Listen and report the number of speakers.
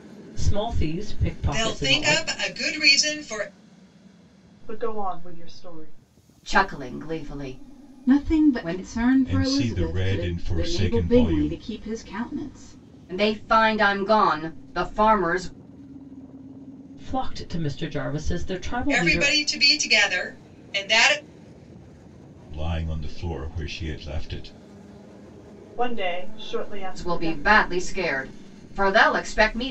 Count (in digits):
6